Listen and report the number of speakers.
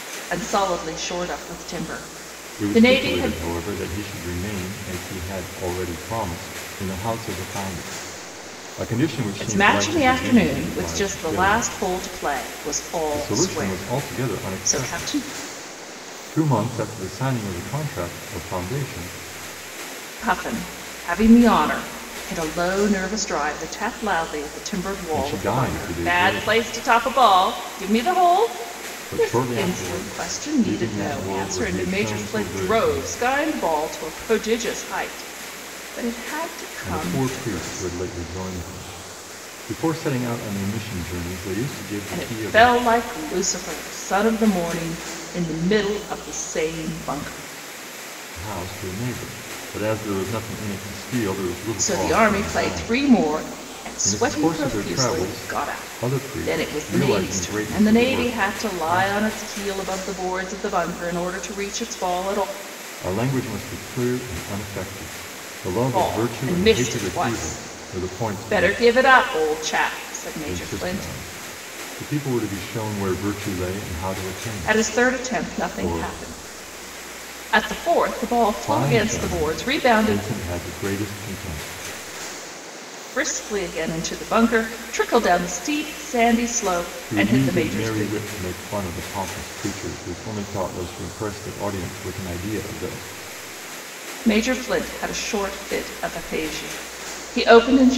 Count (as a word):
two